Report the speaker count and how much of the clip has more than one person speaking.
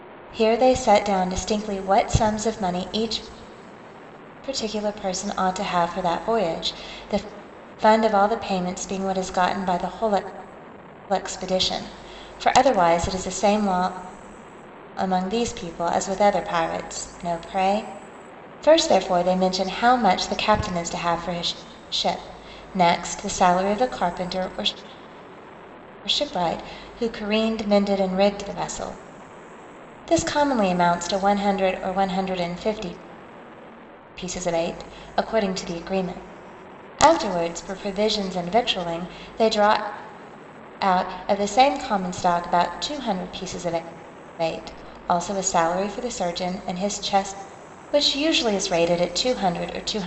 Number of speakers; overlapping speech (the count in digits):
1, no overlap